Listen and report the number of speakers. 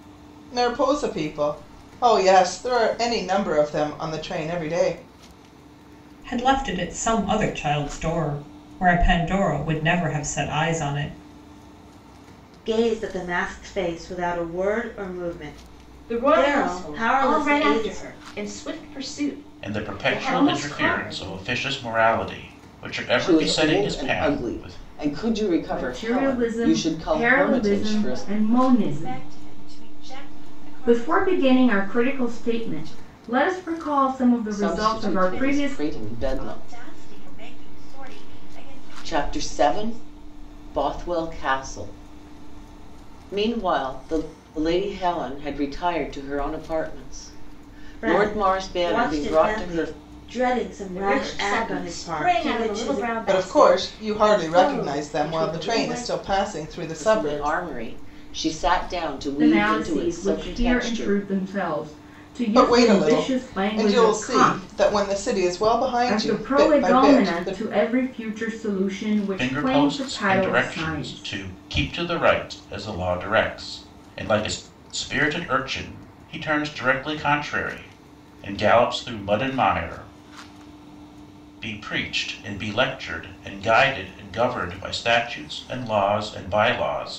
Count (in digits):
8